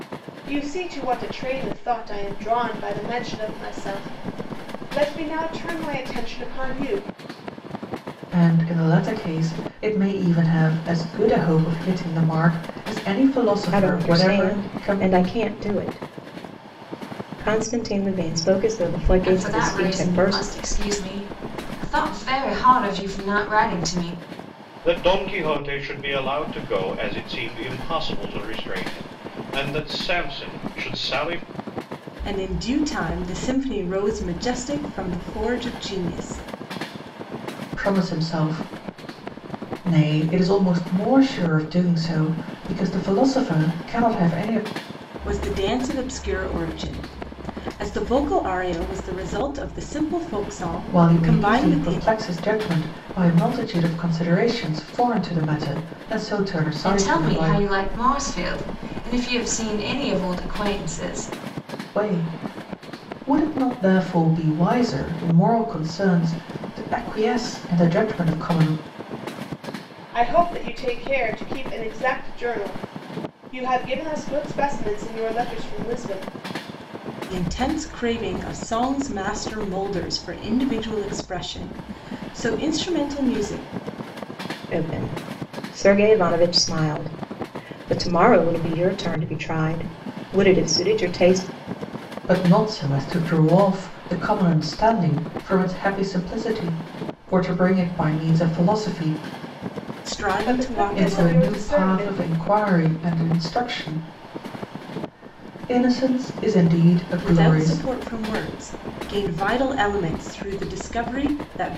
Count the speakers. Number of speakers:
six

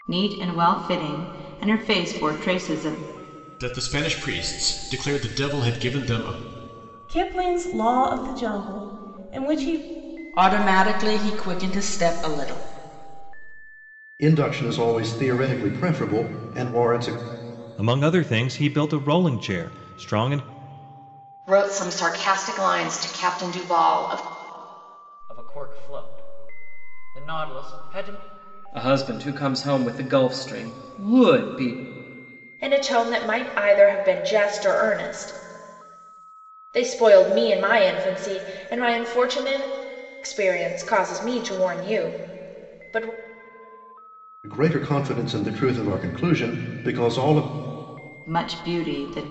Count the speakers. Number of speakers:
ten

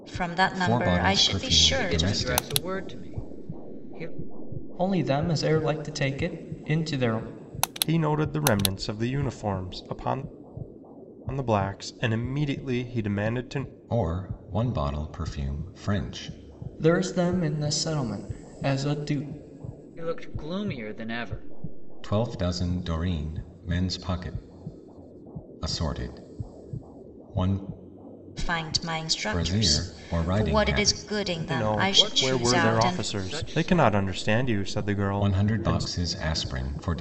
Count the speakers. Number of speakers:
five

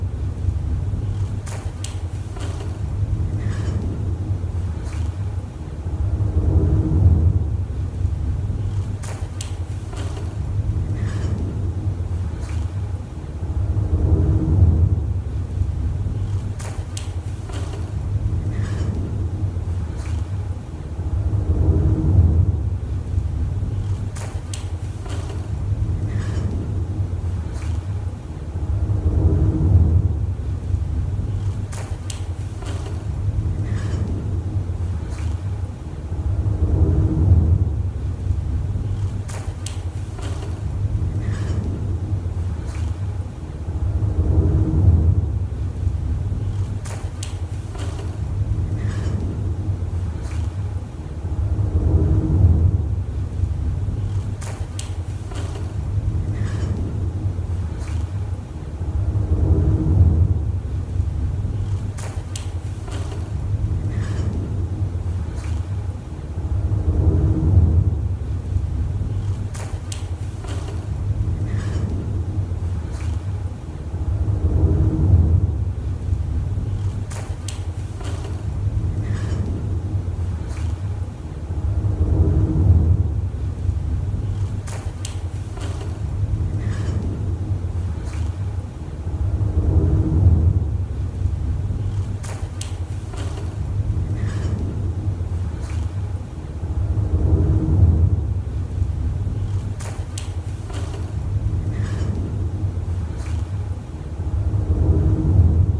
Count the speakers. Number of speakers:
zero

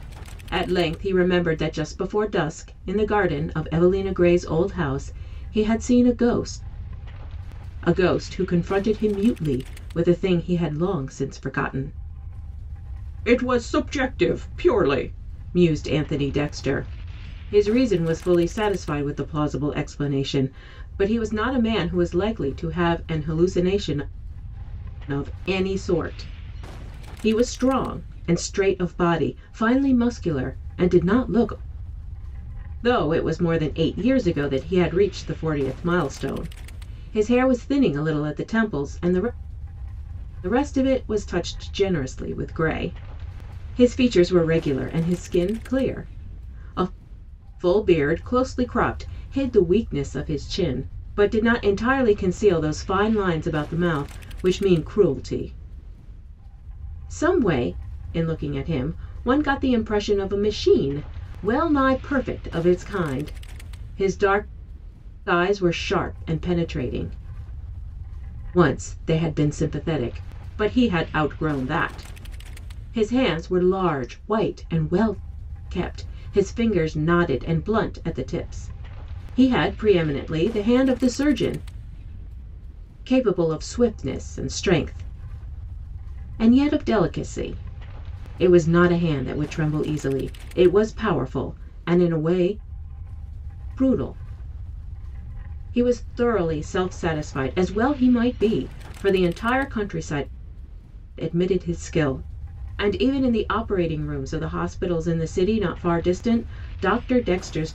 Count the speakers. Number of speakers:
one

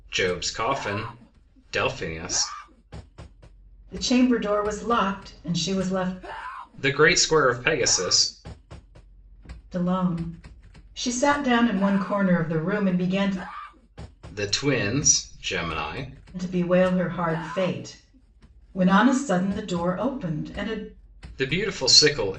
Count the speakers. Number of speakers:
two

